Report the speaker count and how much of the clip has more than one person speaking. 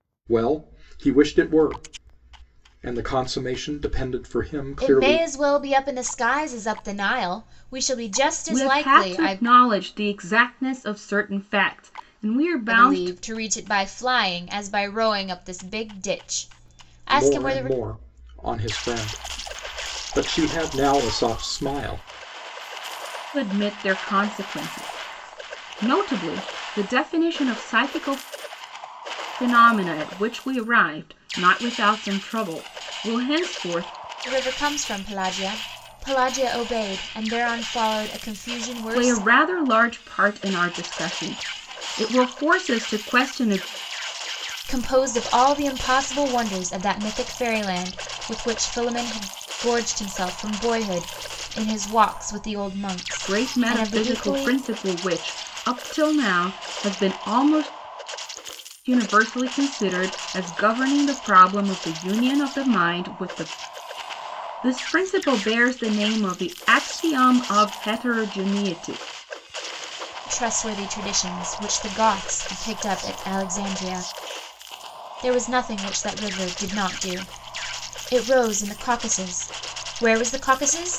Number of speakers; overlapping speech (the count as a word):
three, about 5%